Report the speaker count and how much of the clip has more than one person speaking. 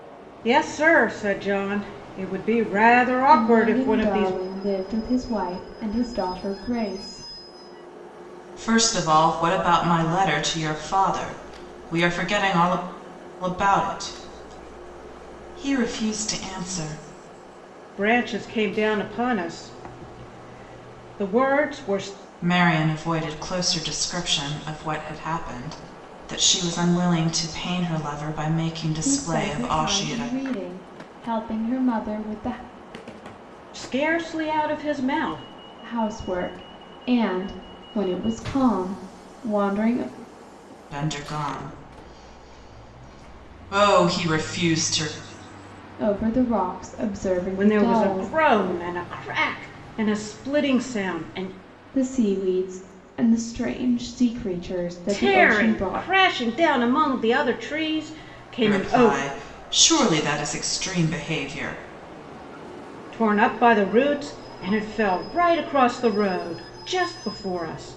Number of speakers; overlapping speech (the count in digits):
3, about 8%